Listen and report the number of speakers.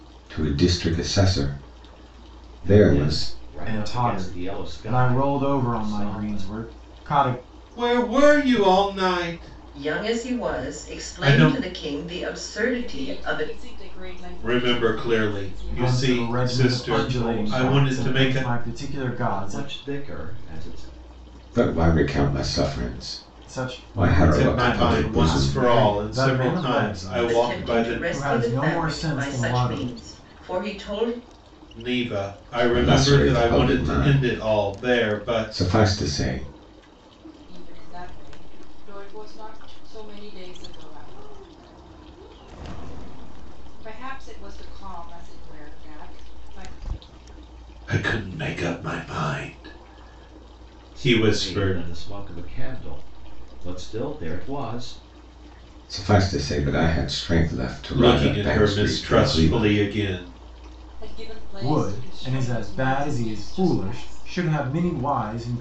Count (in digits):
6